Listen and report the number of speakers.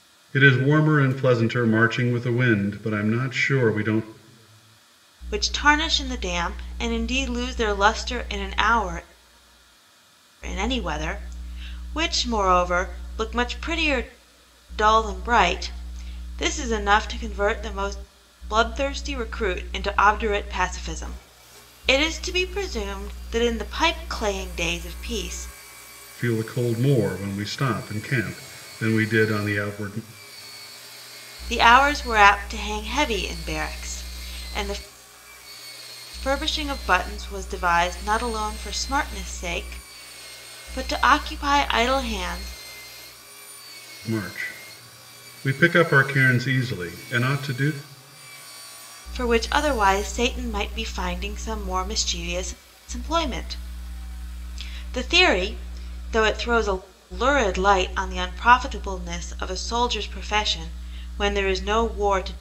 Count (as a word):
two